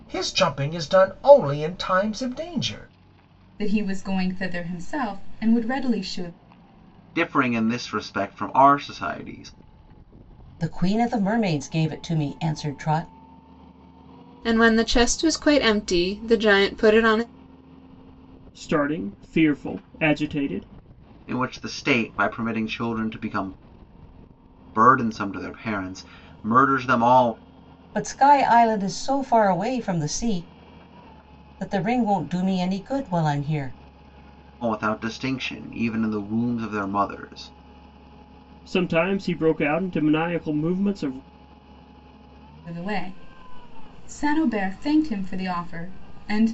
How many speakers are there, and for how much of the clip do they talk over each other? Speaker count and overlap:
6, no overlap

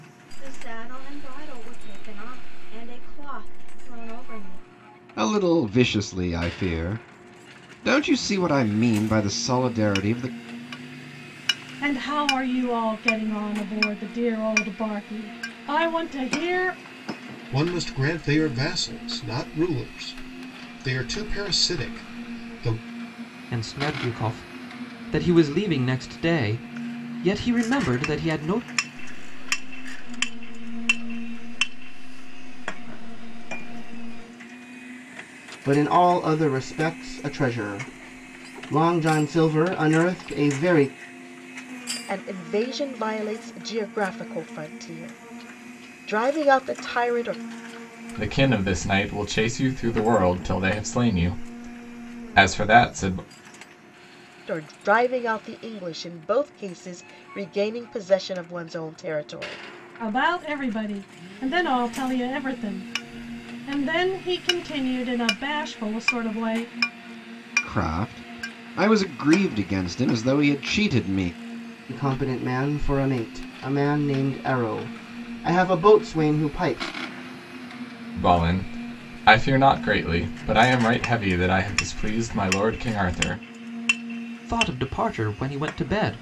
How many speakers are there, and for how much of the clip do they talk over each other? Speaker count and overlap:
9, no overlap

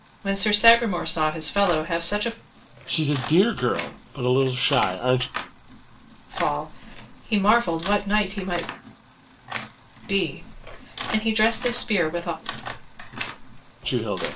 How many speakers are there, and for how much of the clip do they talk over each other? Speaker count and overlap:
2, no overlap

